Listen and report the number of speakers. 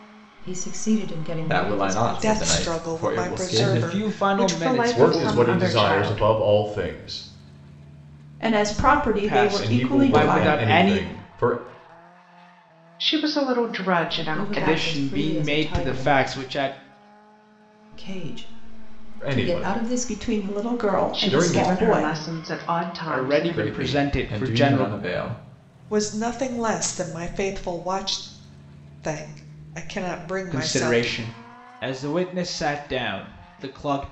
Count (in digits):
7